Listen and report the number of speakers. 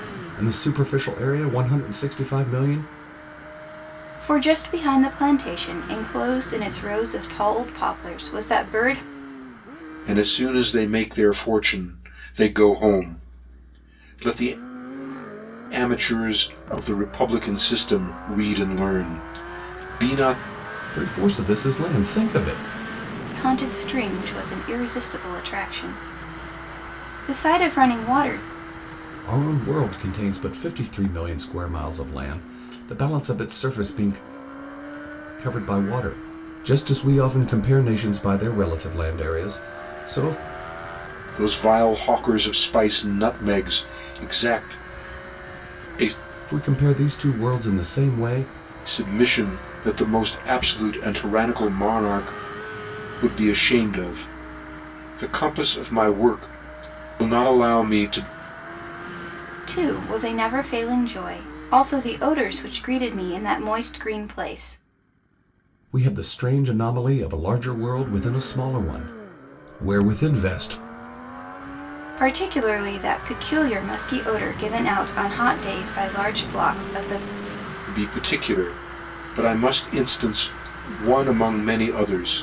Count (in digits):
3